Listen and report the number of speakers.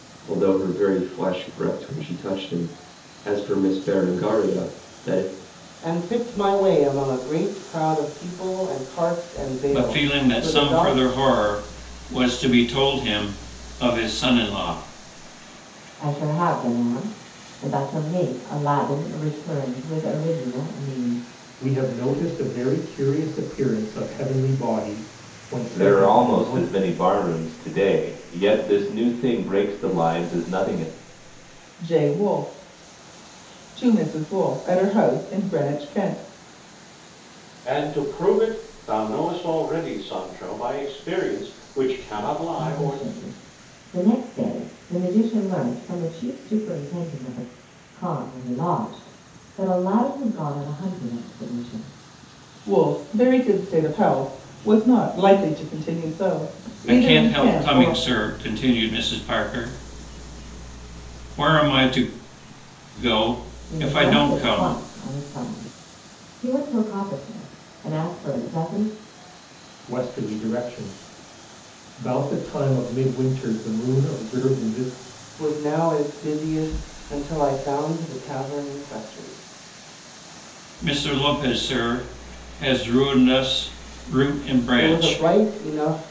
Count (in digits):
8